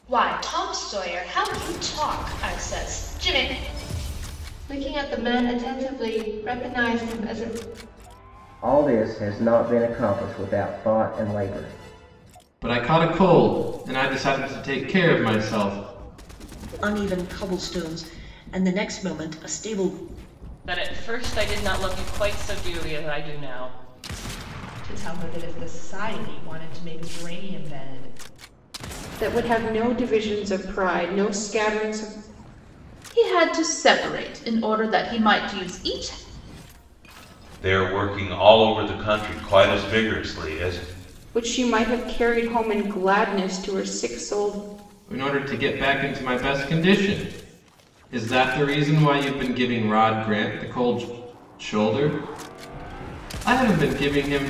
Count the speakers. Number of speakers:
10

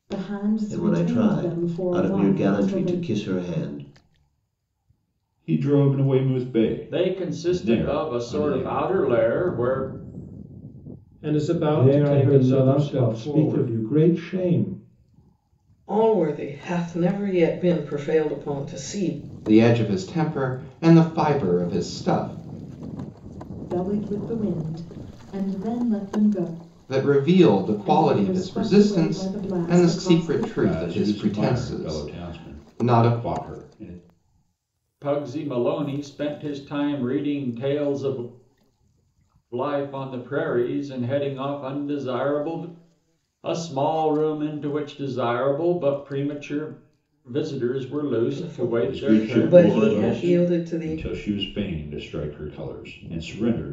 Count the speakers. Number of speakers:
8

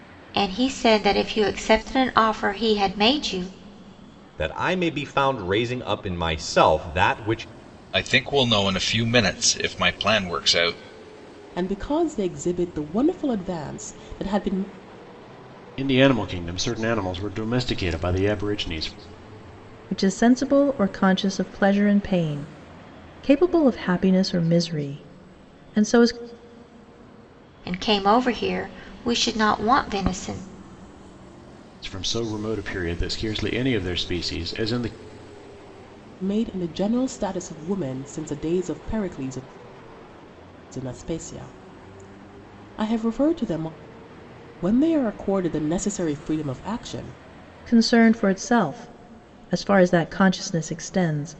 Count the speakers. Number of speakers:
6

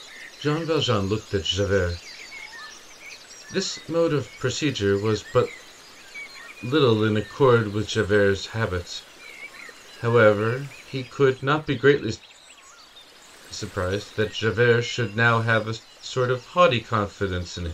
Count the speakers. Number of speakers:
1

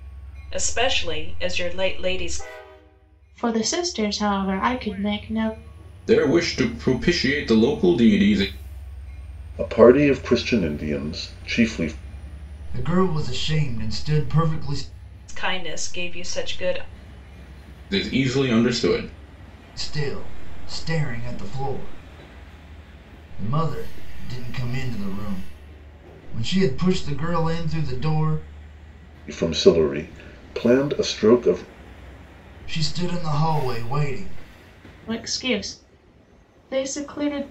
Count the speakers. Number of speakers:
5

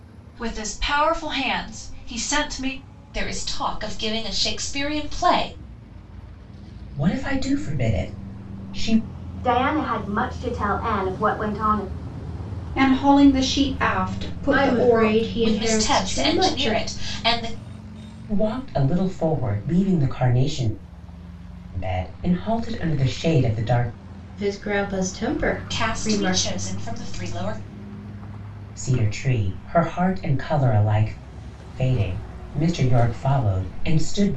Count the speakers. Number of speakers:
6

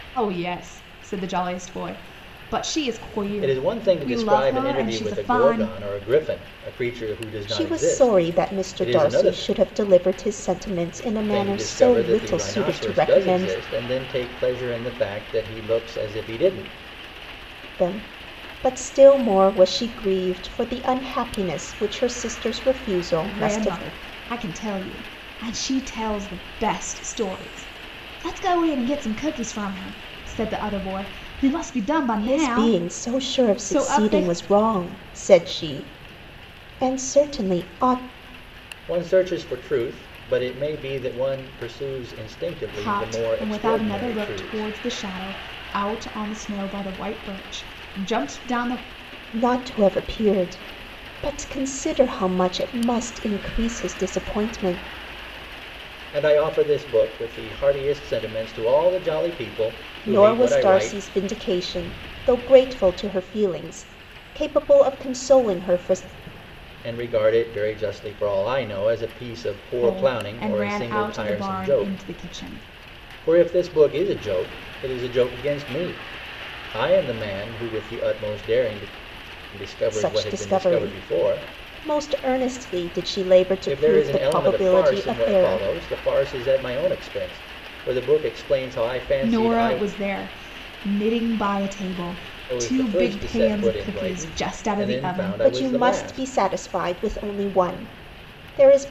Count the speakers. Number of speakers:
3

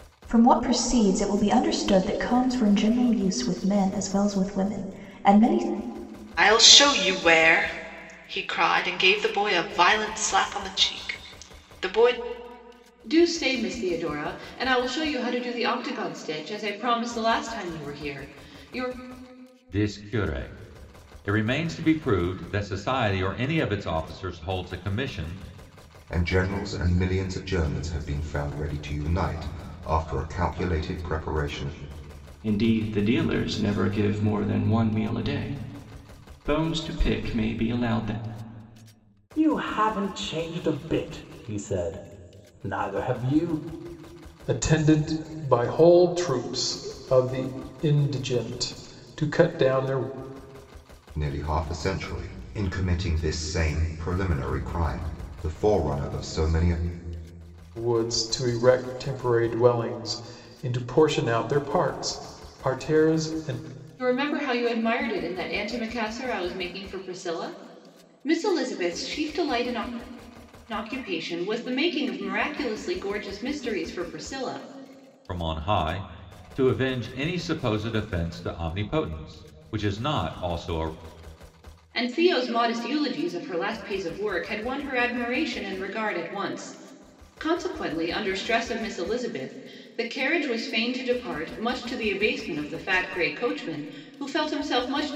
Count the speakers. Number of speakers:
8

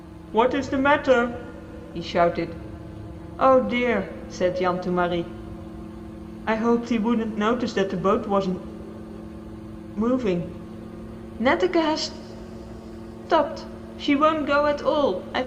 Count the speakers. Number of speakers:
1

